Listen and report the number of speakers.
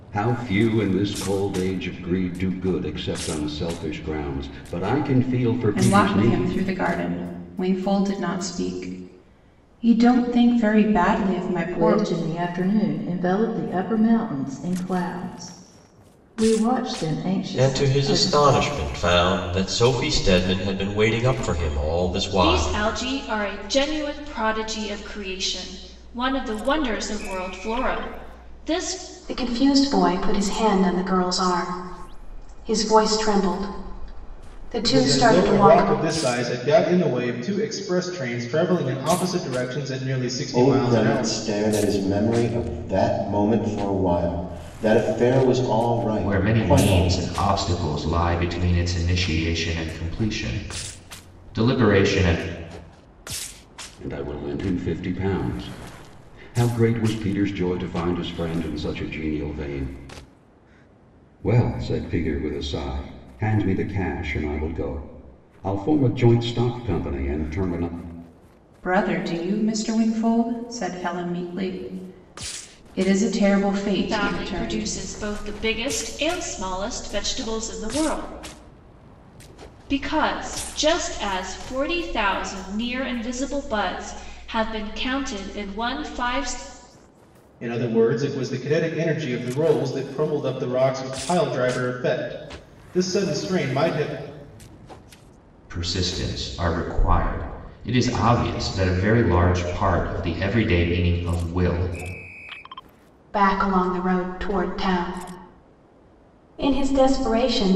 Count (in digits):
9